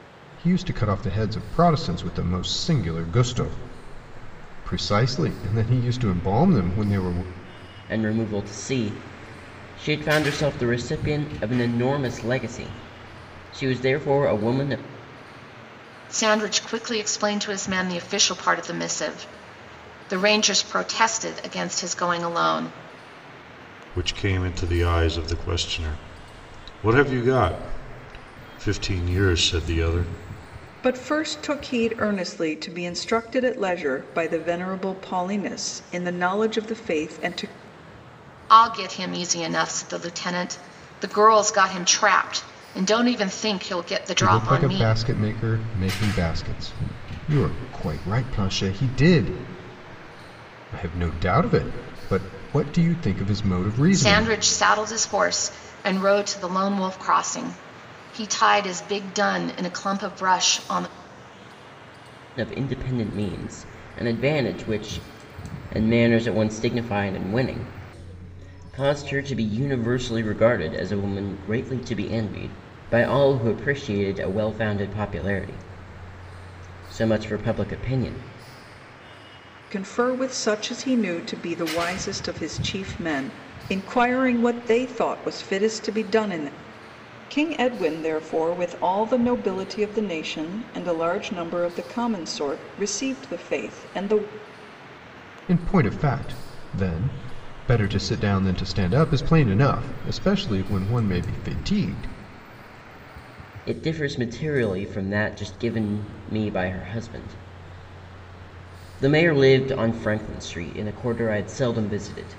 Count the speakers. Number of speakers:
5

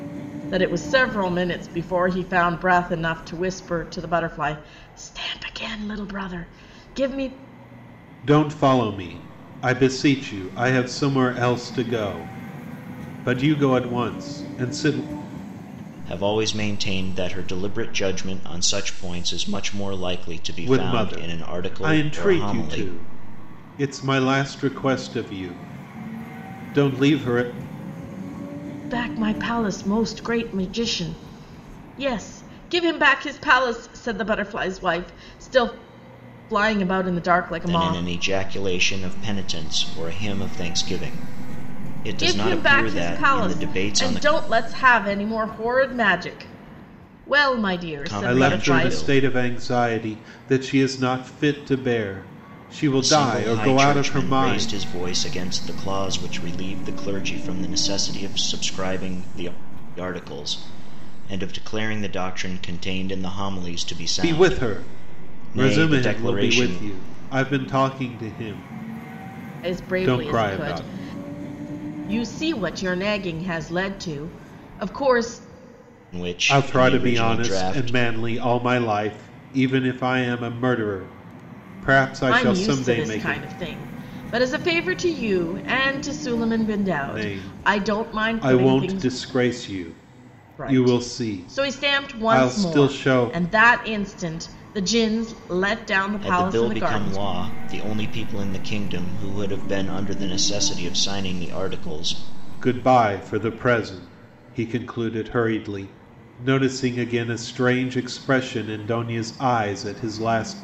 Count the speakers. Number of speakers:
3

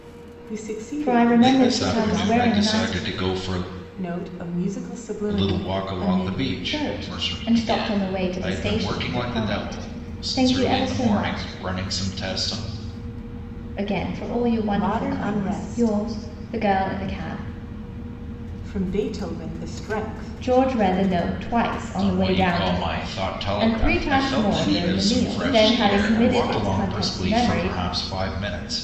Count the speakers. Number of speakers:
3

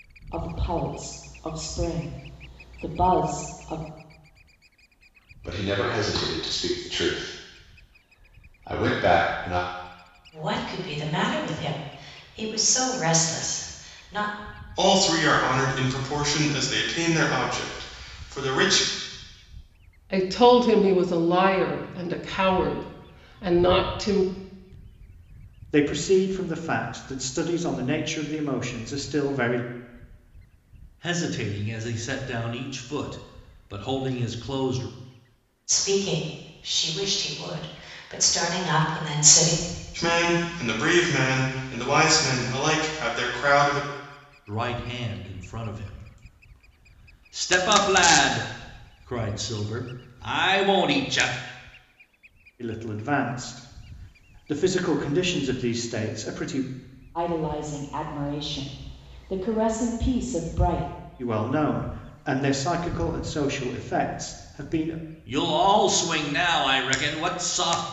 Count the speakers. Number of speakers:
7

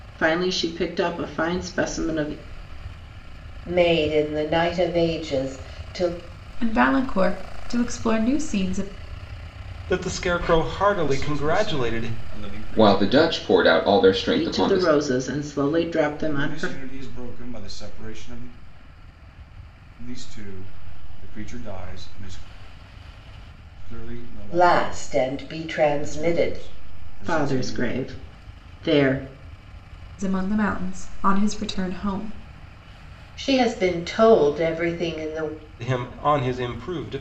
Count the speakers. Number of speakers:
6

